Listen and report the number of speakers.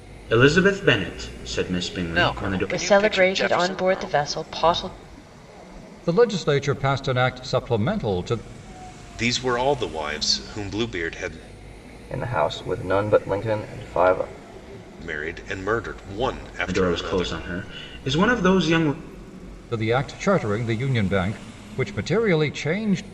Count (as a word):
six